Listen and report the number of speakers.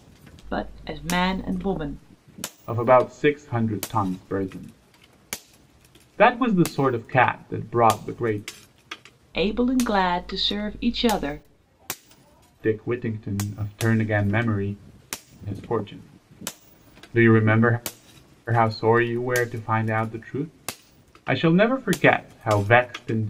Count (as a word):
two